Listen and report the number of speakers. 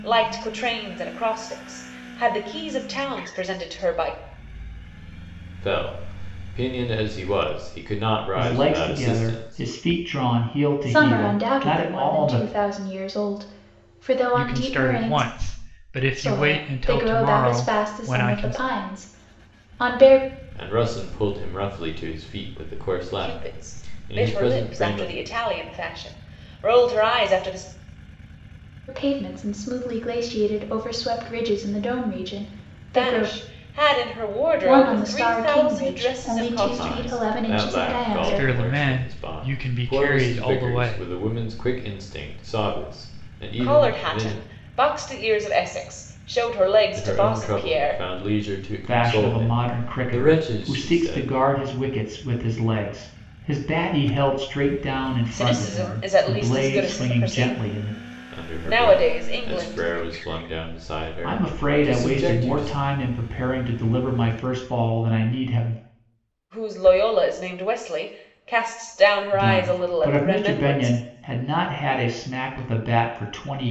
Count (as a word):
five